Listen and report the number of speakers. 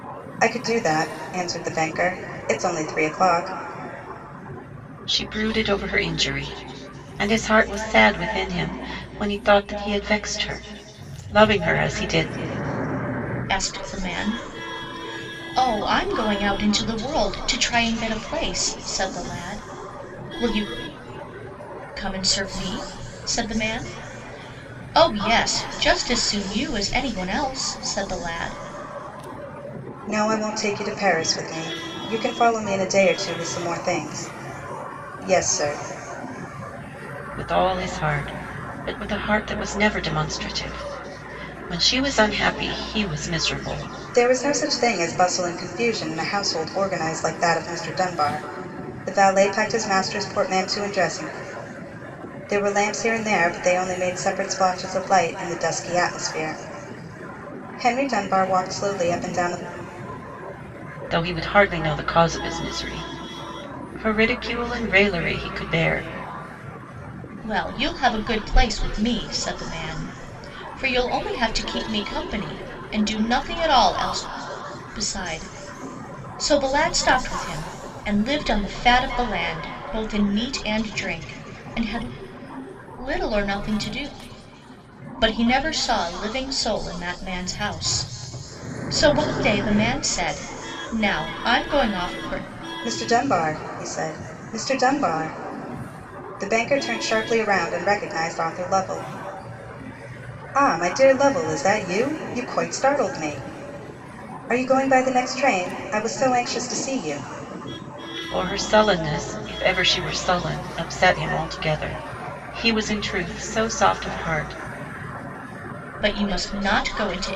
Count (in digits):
3